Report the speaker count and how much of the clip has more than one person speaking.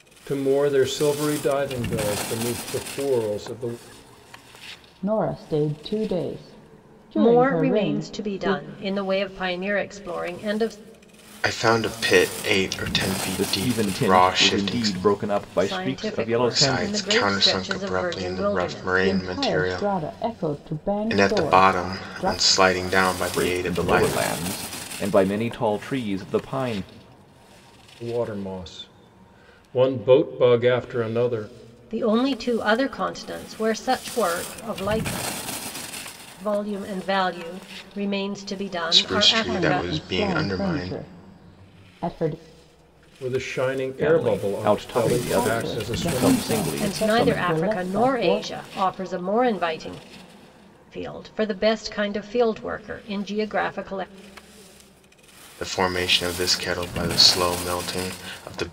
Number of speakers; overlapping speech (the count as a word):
five, about 28%